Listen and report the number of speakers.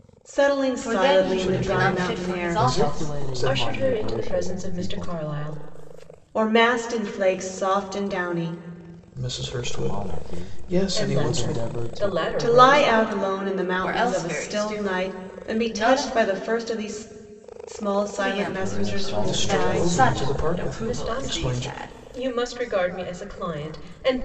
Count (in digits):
5